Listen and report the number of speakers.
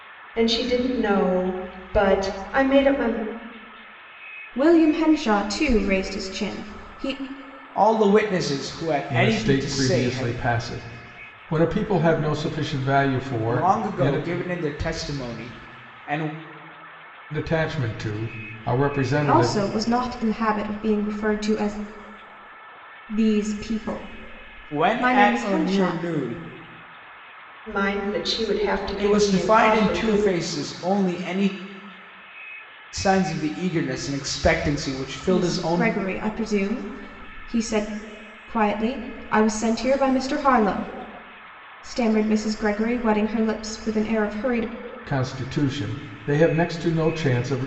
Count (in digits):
4